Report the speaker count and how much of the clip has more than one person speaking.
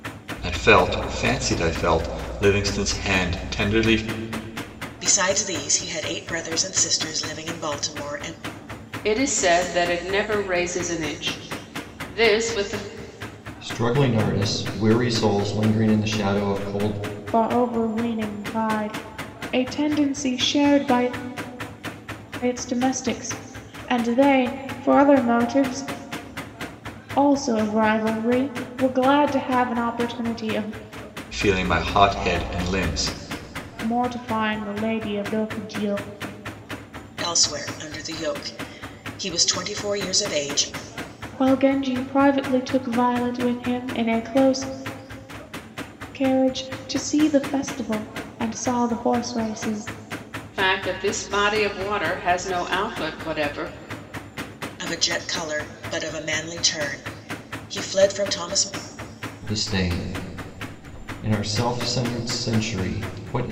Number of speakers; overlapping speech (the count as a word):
five, no overlap